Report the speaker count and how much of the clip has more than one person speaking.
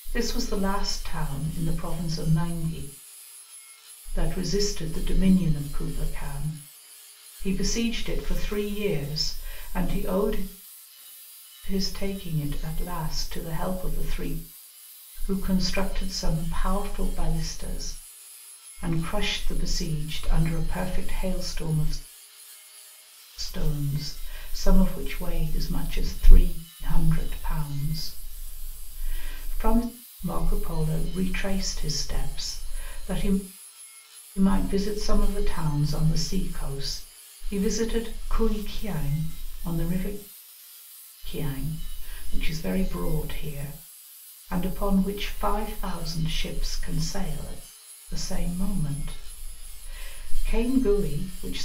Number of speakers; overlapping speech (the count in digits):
1, no overlap